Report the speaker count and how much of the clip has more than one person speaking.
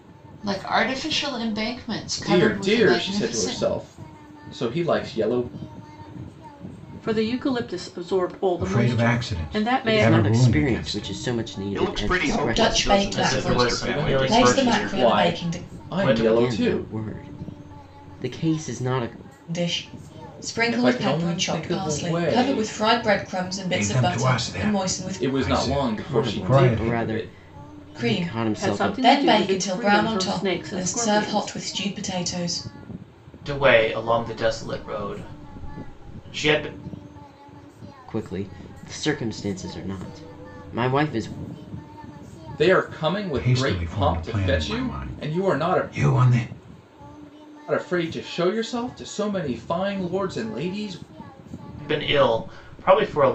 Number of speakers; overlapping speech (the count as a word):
eight, about 40%